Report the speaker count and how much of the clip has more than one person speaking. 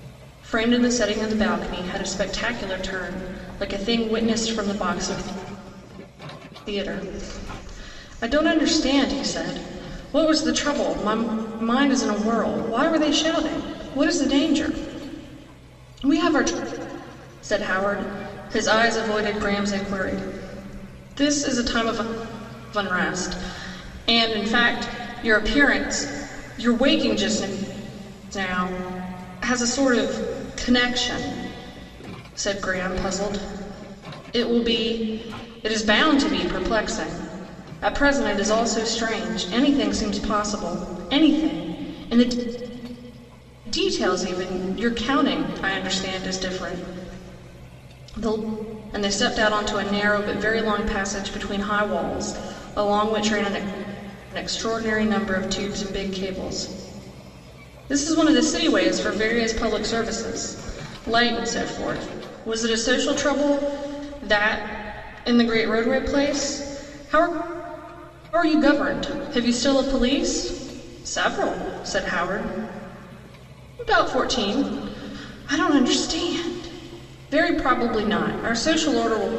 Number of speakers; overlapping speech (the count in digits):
1, no overlap